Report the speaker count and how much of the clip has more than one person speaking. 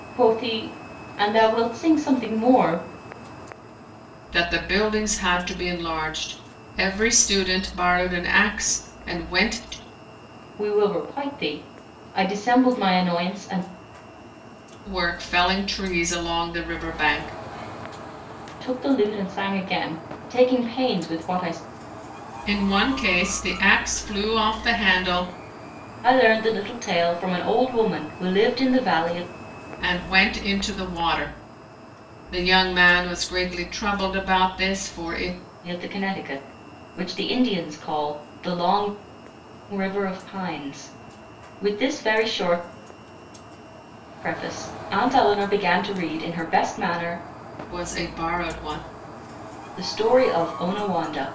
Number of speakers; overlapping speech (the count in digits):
2, no overlap